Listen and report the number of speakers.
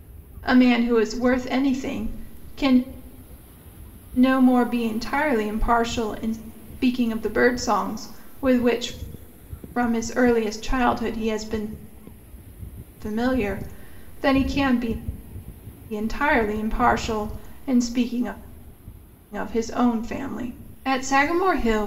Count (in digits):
1